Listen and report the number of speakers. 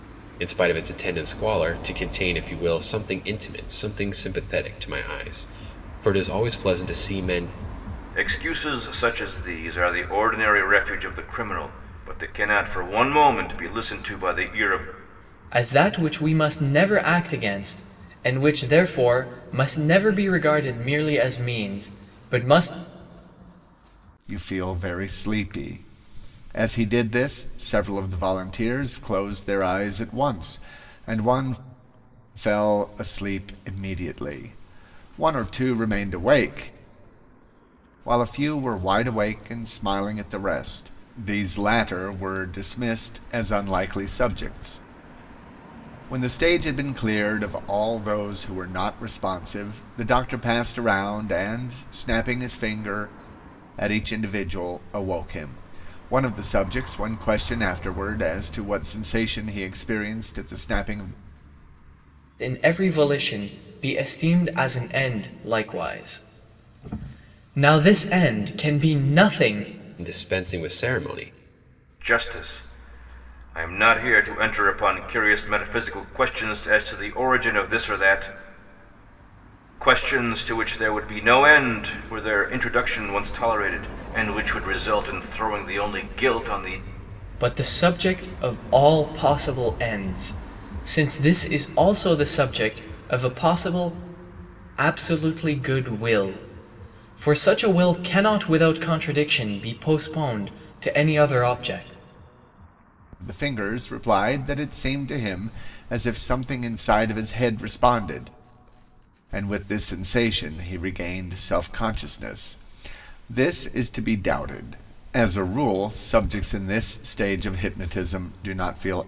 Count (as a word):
four